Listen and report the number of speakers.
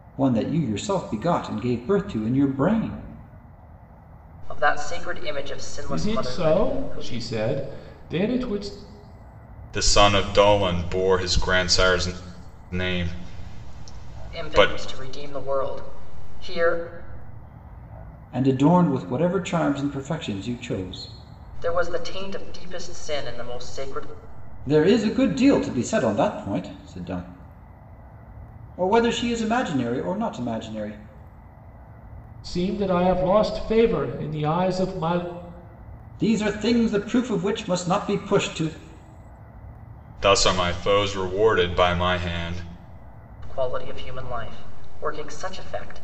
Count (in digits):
4